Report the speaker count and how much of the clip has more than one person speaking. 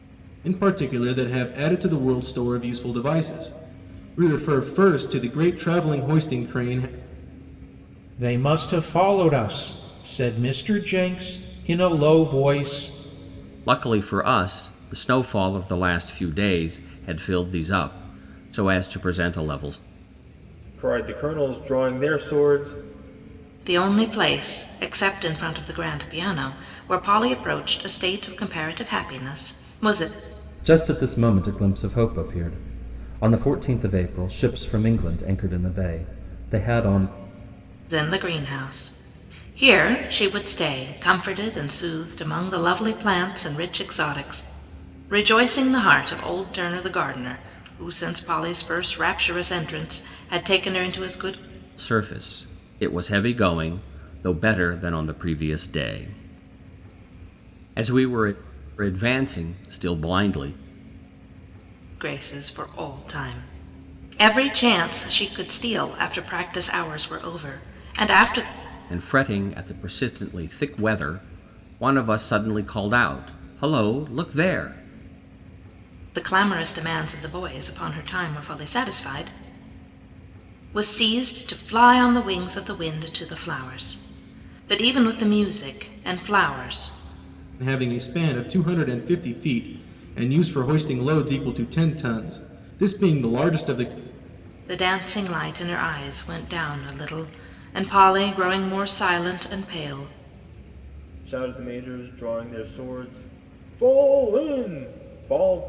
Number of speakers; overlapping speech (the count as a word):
six, no overlap